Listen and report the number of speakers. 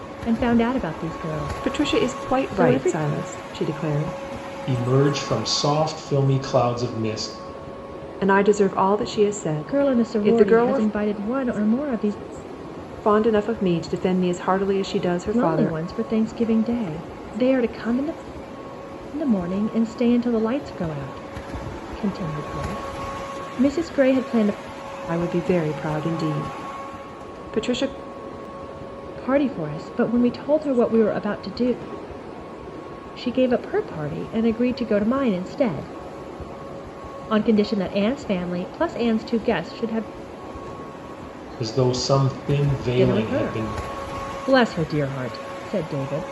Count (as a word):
three